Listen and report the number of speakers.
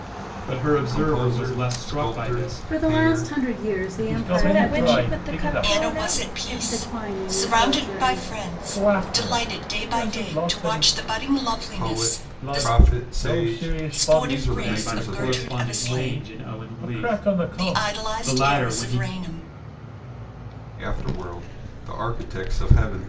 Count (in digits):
6